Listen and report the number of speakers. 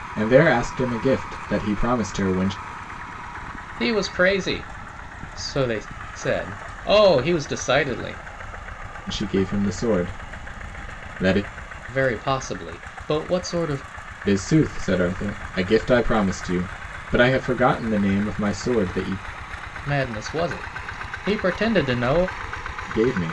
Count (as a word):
two